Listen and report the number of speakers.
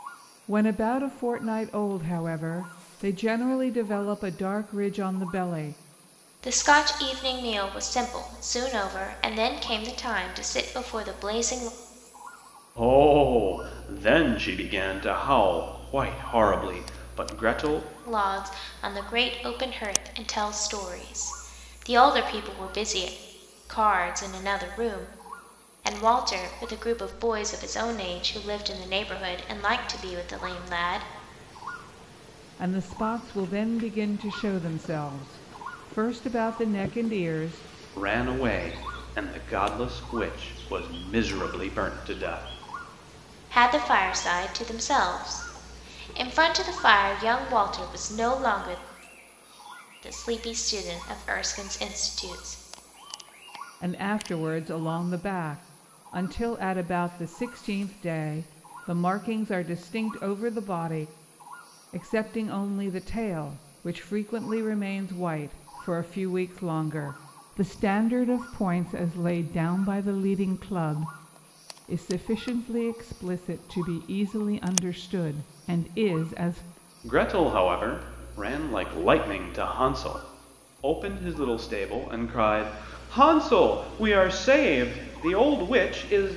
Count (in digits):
3